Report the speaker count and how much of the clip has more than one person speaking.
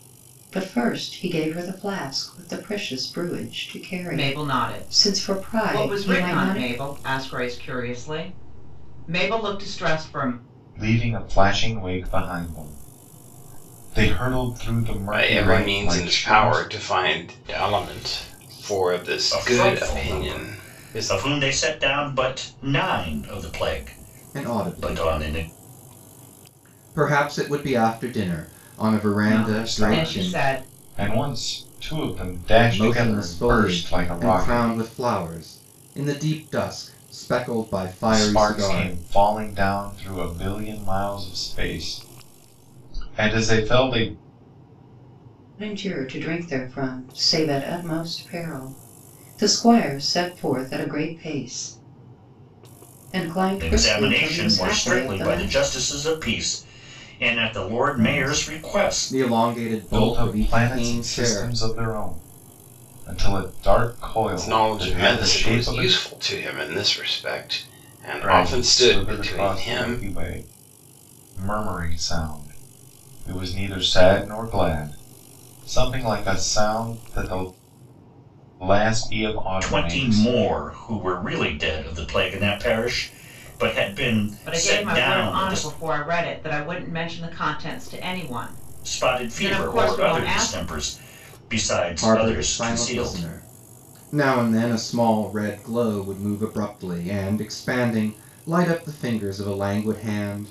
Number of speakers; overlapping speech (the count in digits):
6, about 25%